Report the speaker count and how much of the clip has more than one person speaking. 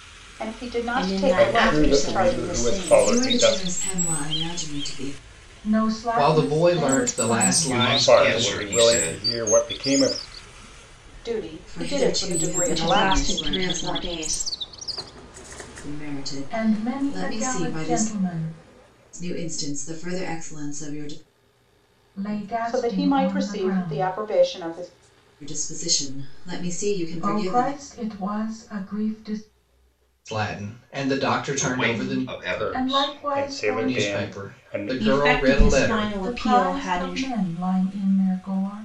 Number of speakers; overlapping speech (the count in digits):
7, about 46%